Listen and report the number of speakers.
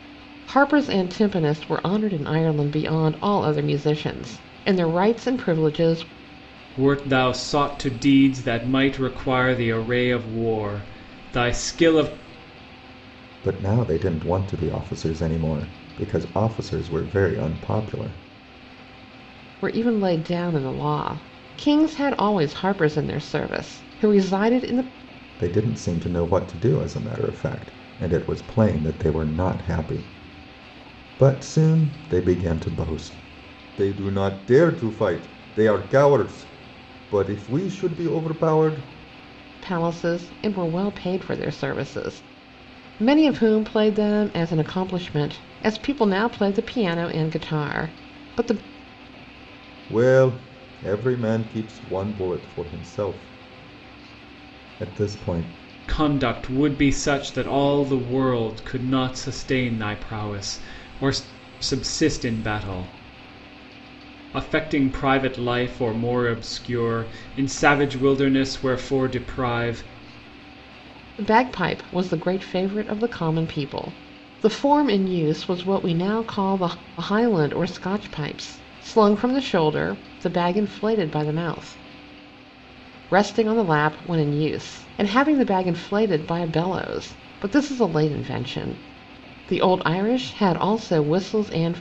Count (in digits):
3